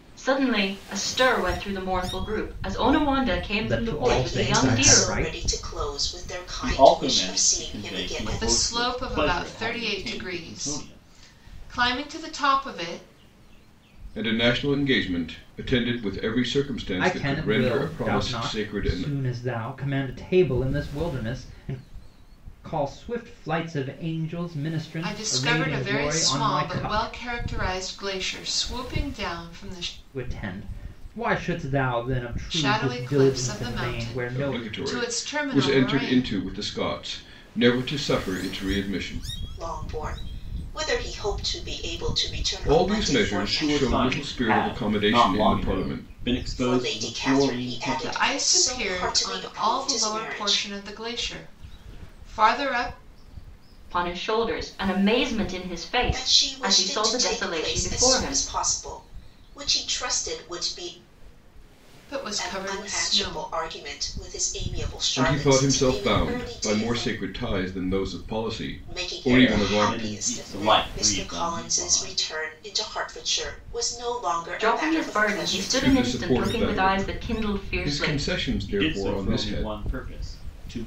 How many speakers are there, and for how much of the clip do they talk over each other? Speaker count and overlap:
six, about 44%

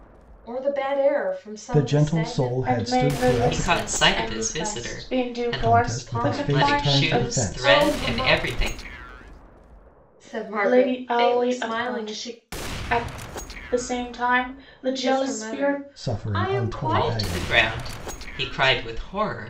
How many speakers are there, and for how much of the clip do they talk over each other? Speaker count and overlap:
four, about 56%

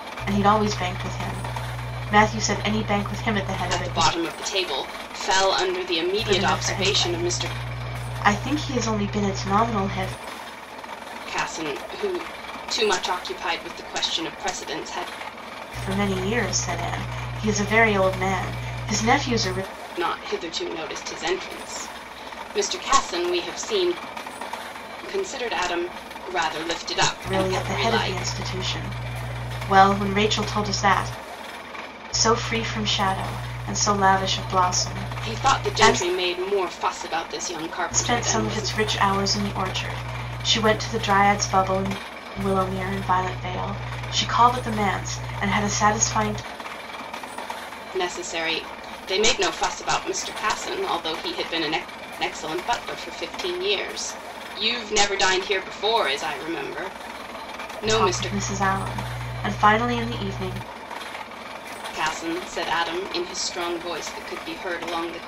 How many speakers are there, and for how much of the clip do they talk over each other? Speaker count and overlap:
two, about 8%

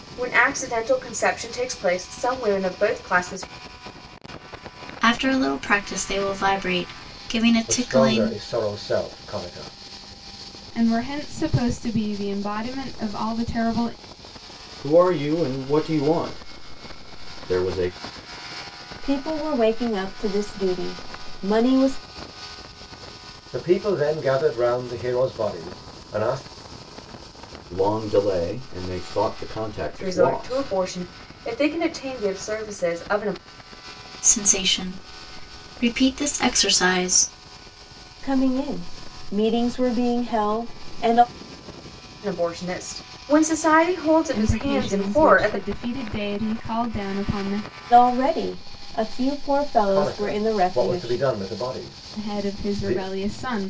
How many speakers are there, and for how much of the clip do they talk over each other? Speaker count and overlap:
six, about 9%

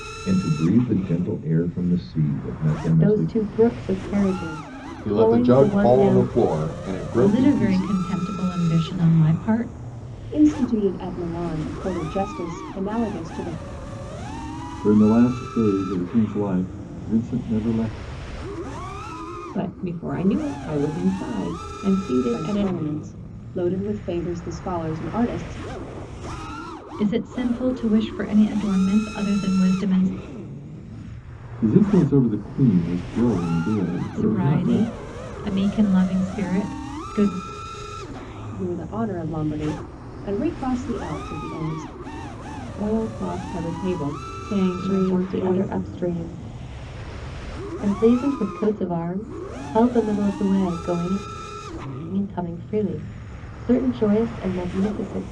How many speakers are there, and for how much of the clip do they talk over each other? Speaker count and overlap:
seven, about 10%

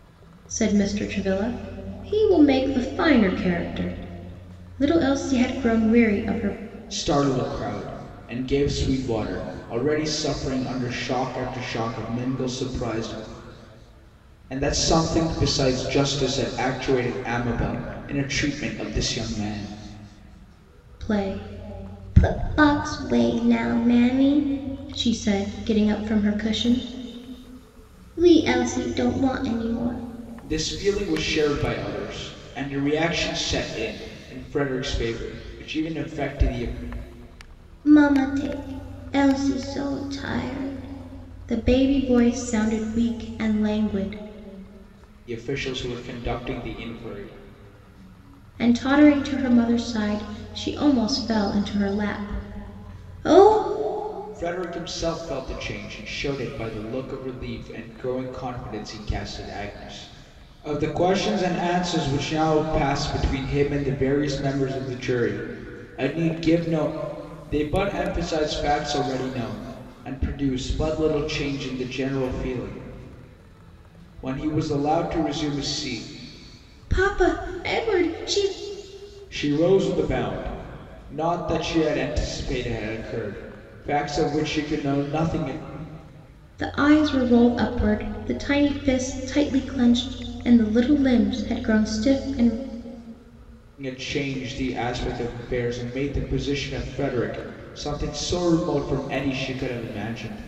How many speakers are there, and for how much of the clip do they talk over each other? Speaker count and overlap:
two, no overlap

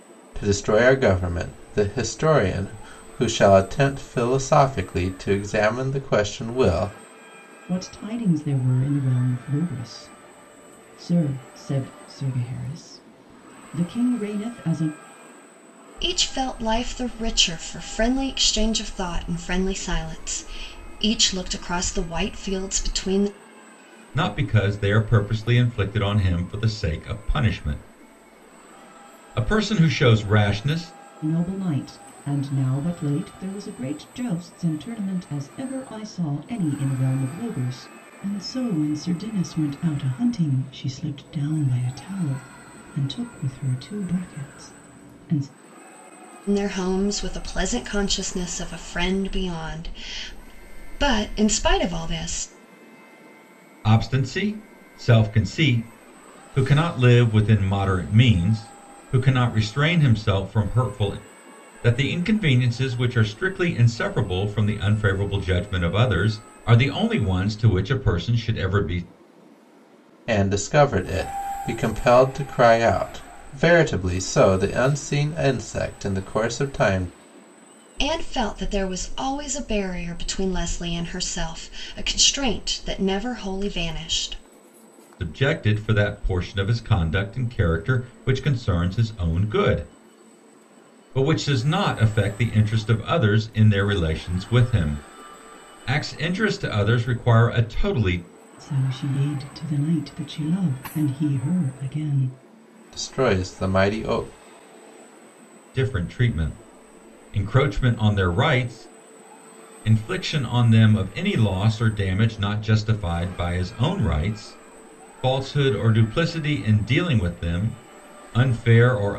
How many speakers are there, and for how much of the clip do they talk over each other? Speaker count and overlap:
four, no overlap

